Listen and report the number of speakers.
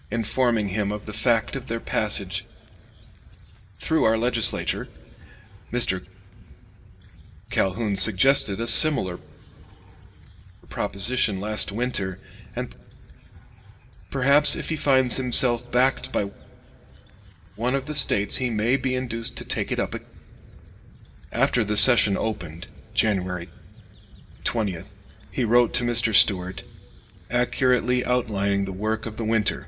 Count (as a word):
one